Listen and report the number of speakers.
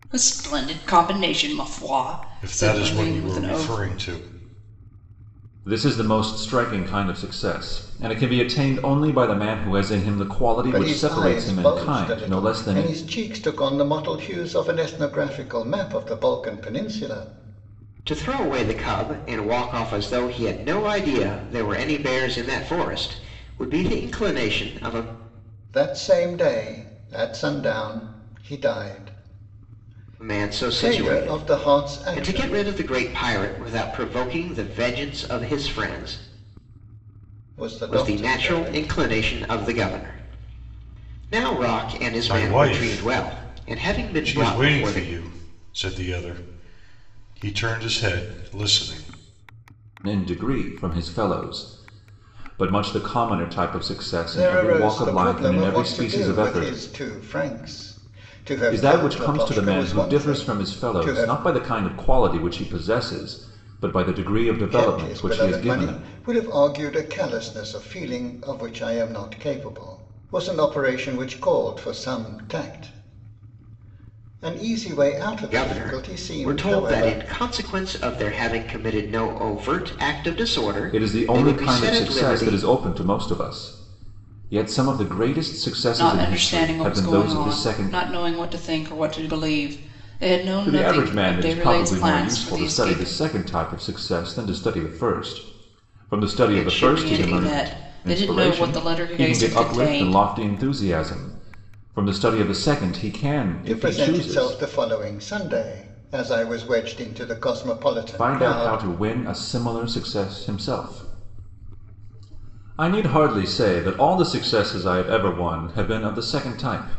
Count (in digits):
5